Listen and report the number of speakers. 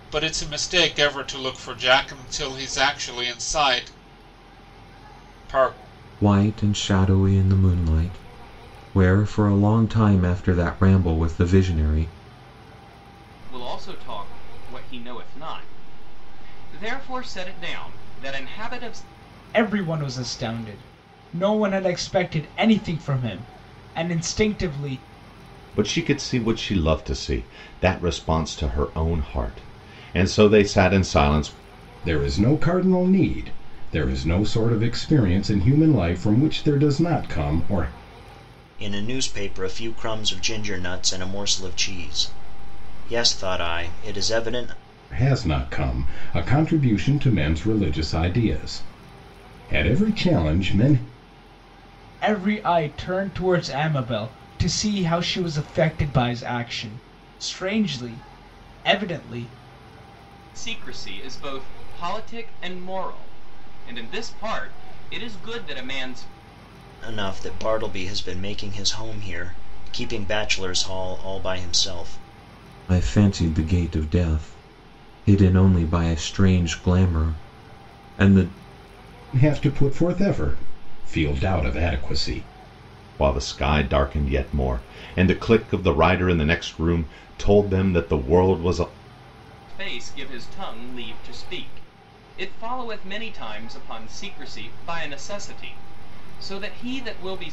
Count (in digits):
7